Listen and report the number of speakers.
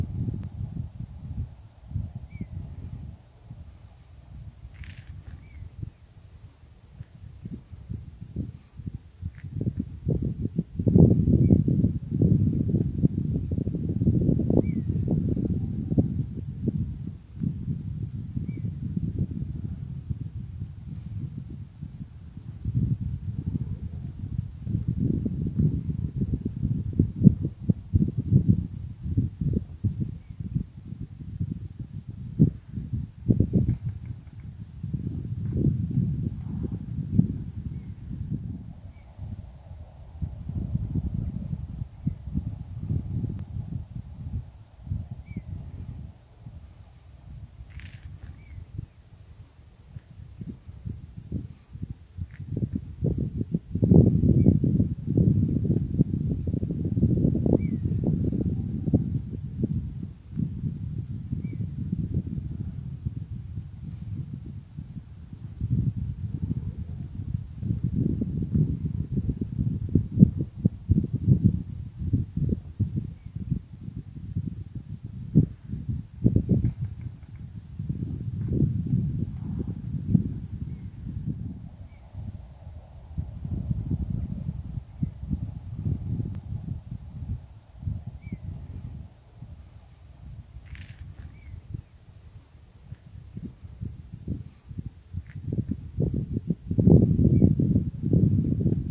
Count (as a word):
zero